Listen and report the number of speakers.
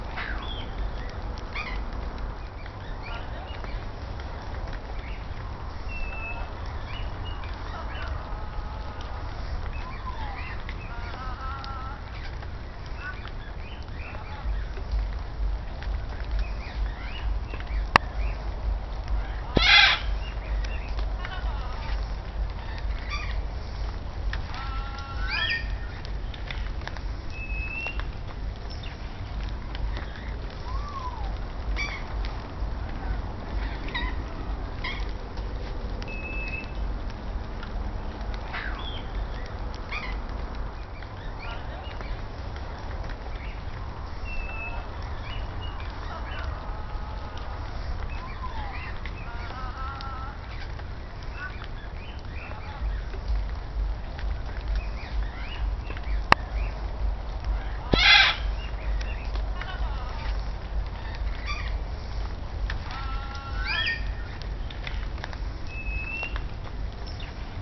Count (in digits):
0